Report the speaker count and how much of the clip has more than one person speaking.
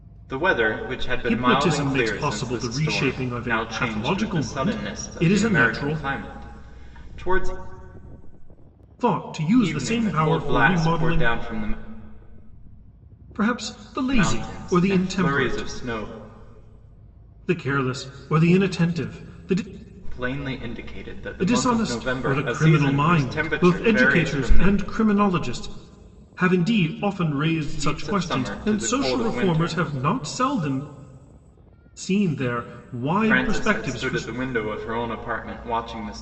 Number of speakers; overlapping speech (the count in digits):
2, about 41%